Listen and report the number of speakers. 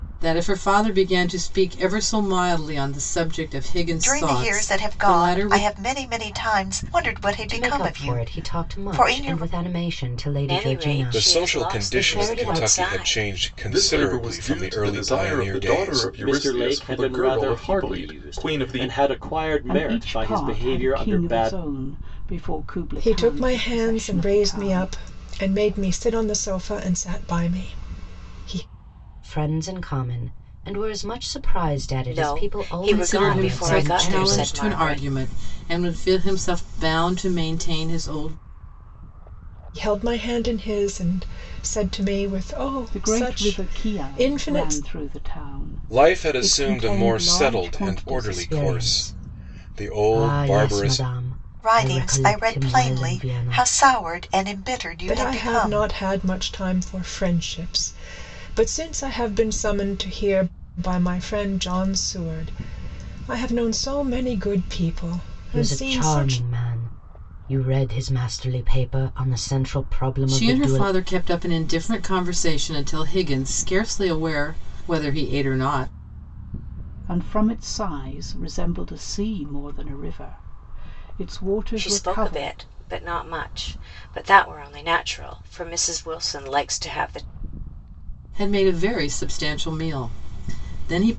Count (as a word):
nine